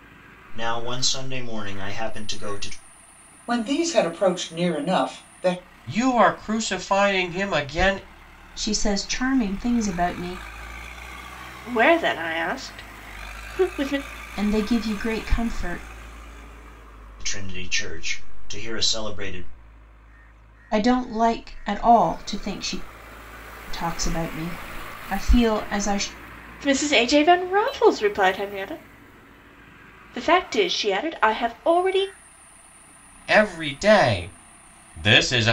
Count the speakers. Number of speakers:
5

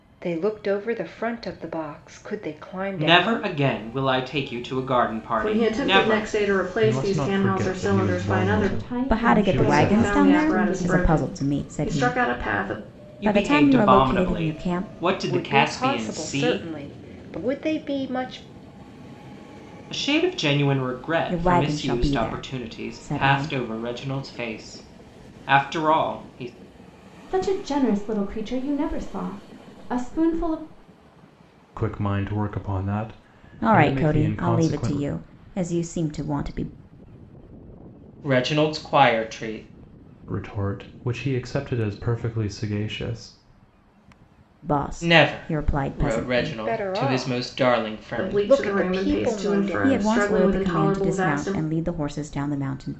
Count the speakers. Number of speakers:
6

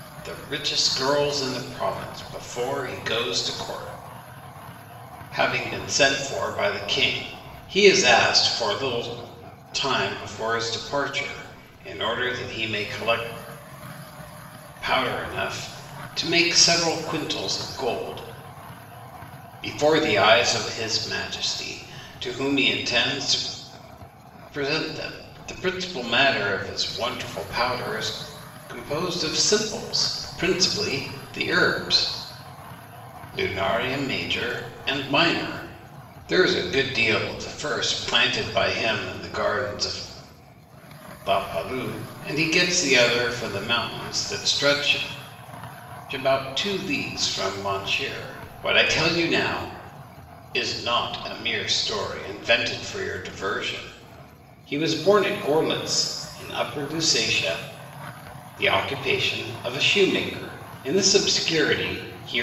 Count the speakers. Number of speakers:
1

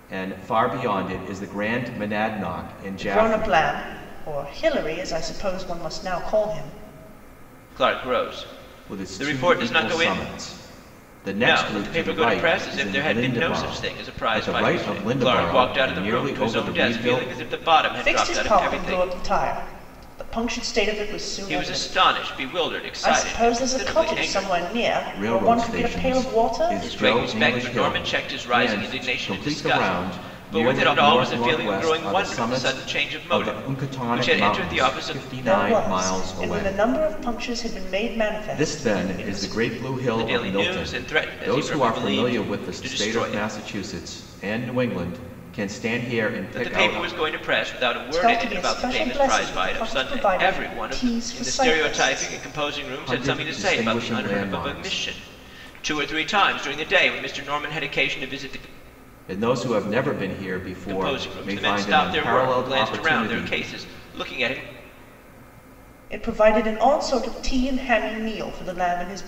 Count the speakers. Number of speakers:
3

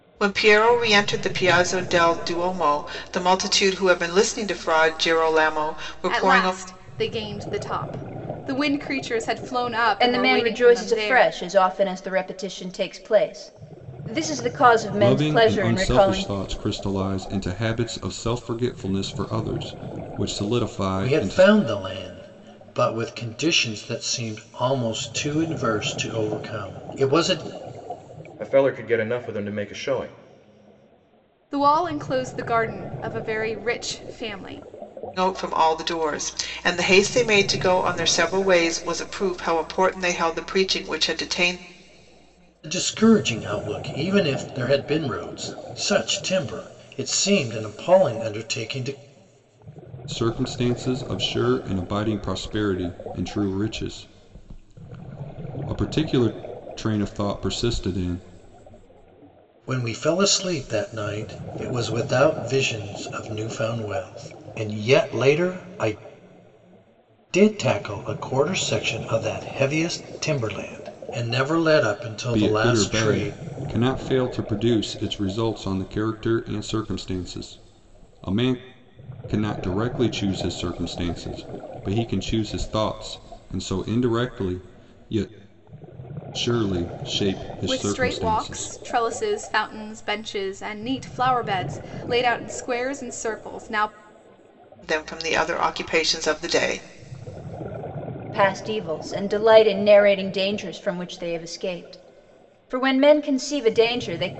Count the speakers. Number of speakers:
6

